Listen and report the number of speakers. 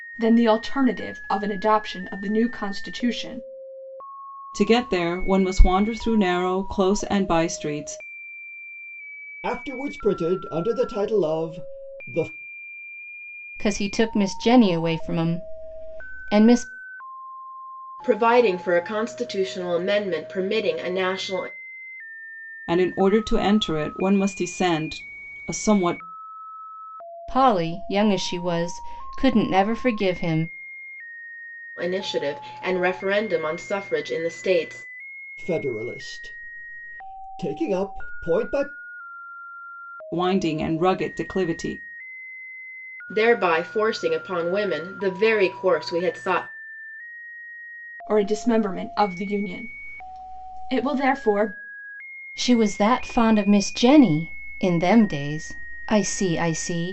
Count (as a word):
five